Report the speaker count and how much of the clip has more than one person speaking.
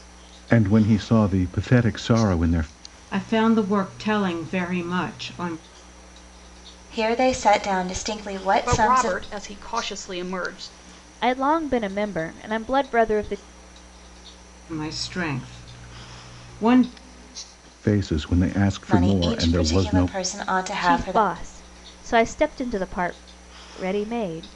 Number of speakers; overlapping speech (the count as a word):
five, about 10%